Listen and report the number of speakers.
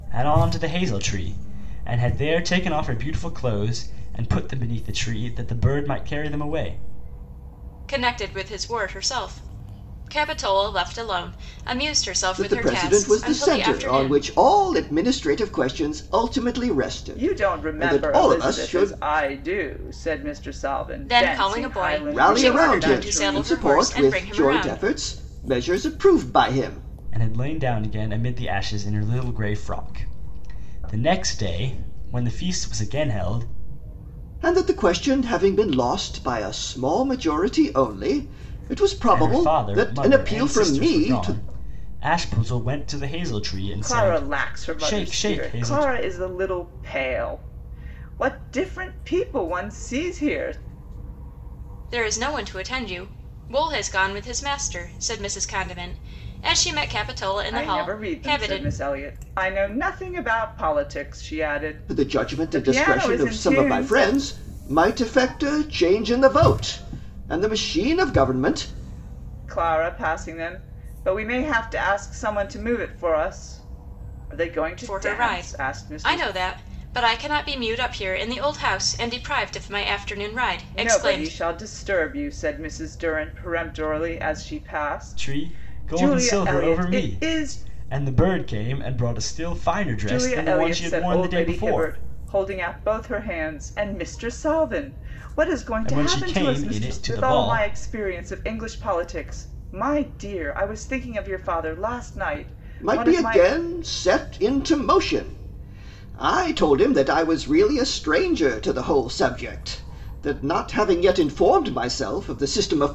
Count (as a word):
four